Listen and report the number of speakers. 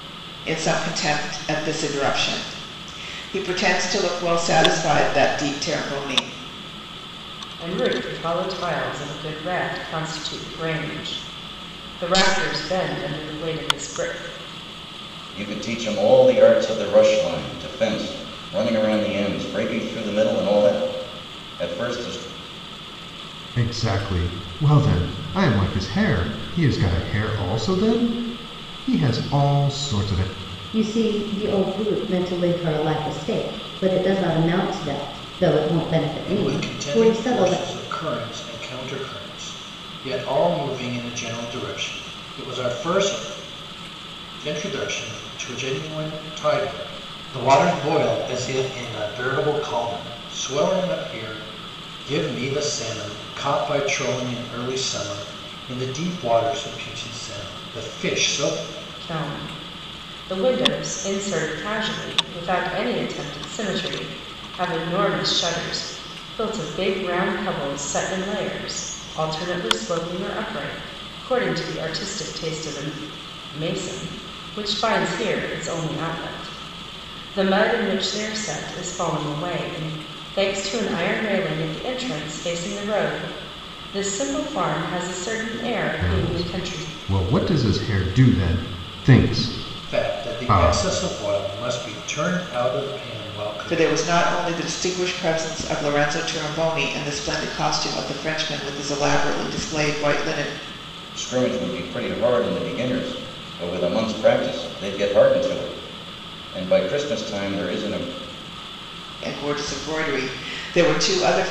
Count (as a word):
six